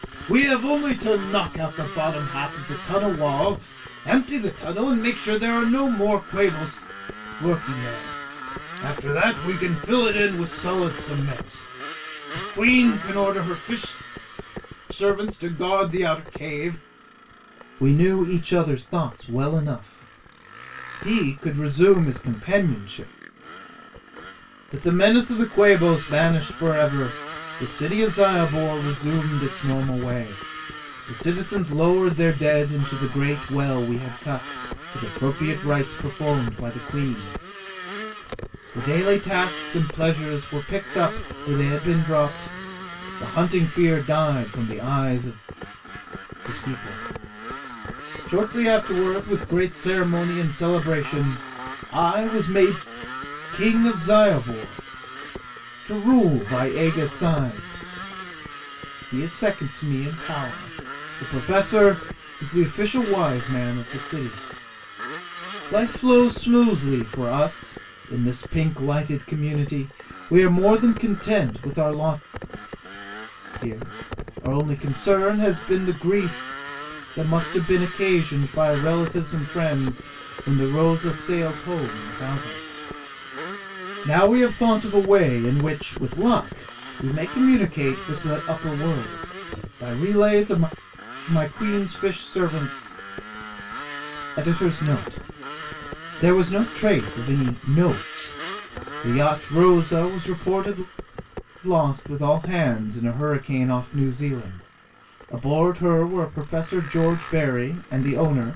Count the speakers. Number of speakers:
one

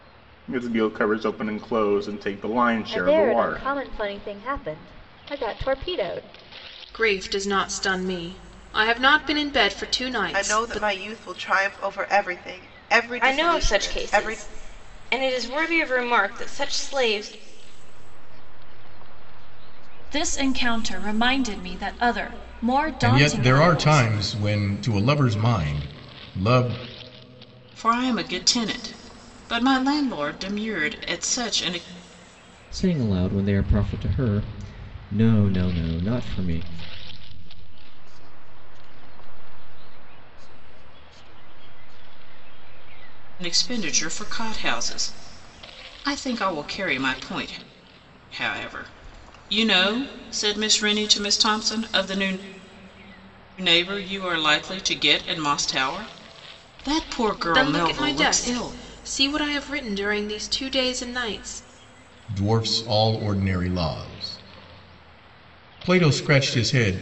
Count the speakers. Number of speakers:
ten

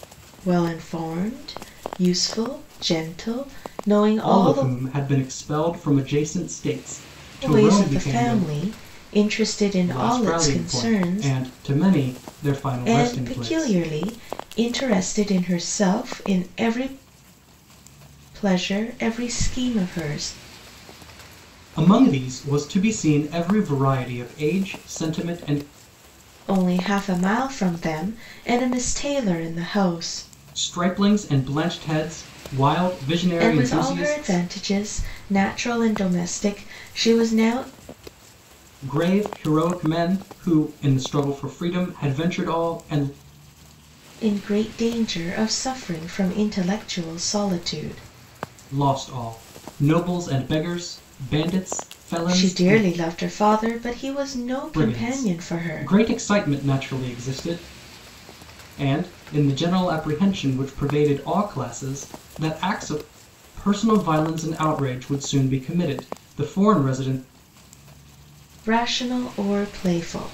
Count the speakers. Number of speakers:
two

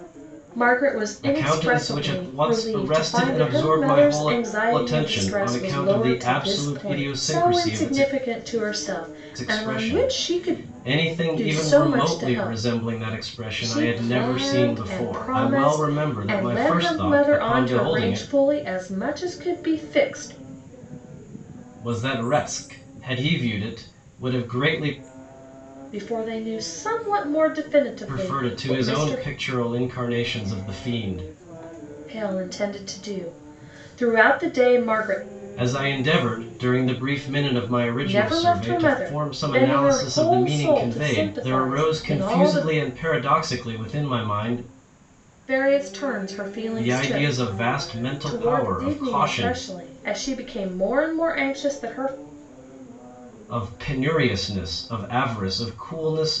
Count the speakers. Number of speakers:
two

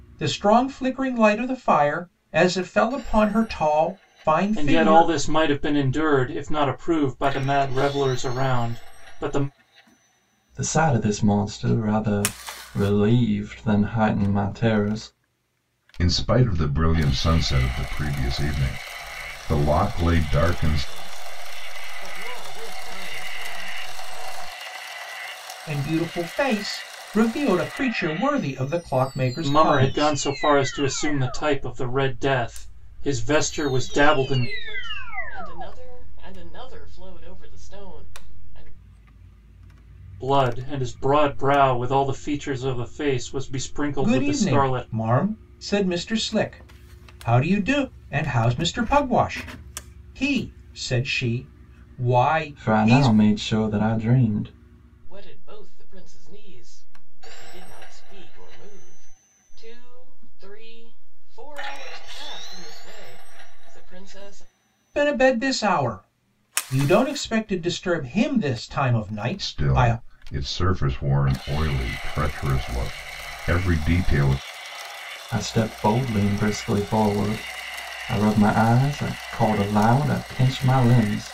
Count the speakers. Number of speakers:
five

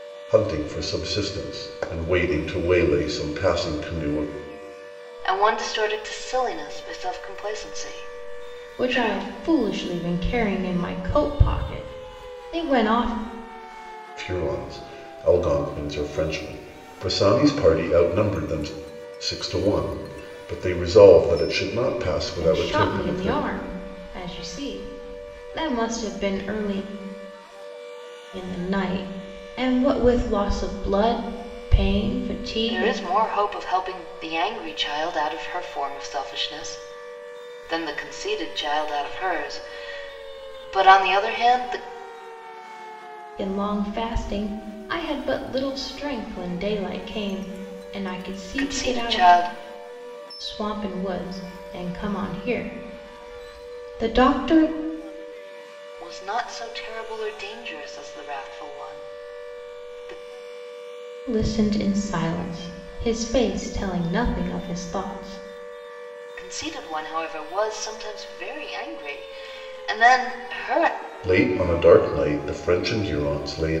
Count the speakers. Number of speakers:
three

